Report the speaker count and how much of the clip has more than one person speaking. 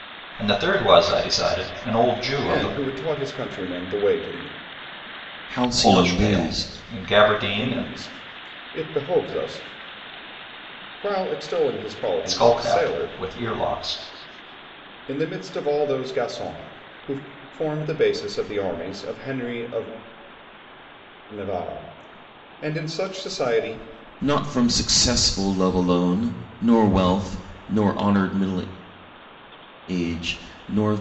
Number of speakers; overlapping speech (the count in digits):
3, about 9%